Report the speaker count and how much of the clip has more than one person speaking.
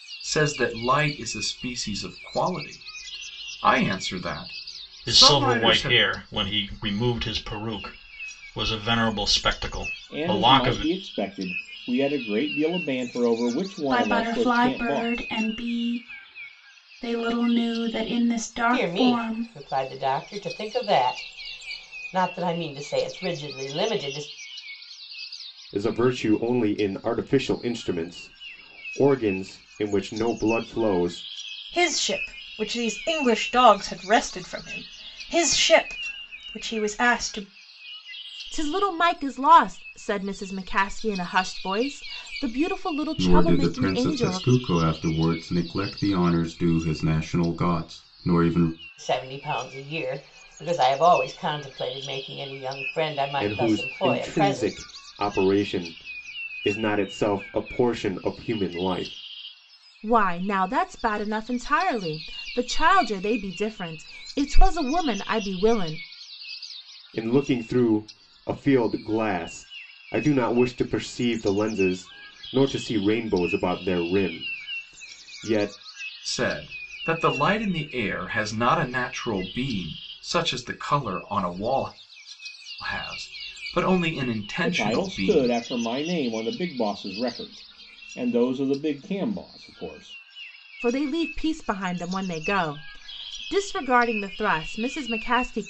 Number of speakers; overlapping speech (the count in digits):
9, about 8%